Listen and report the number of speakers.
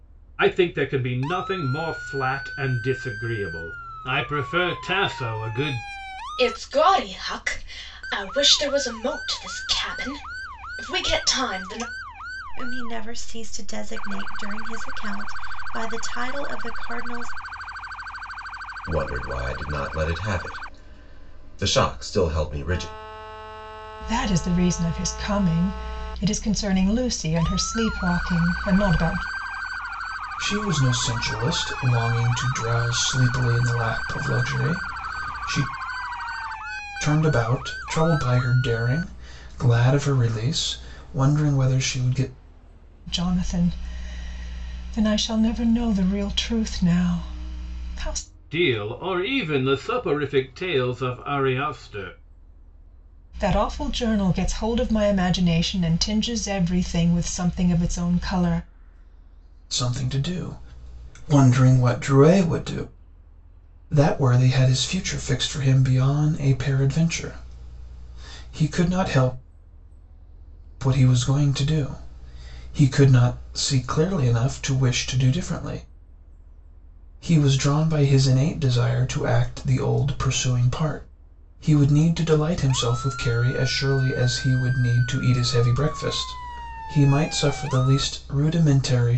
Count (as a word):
six